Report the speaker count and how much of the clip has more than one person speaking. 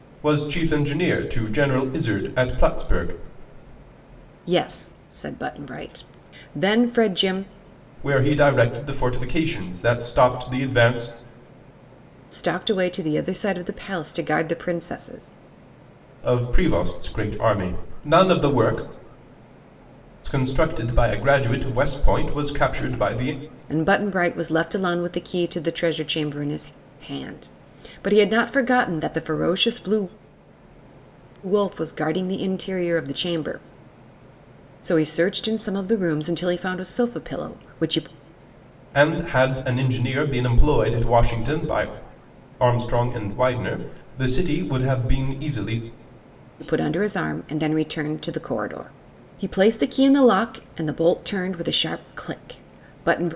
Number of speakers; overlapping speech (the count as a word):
two, no overlap